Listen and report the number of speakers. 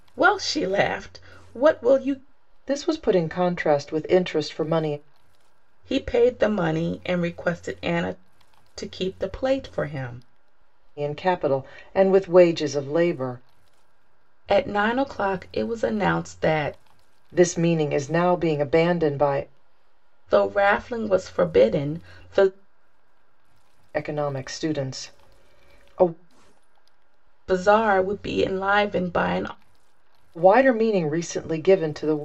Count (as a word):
two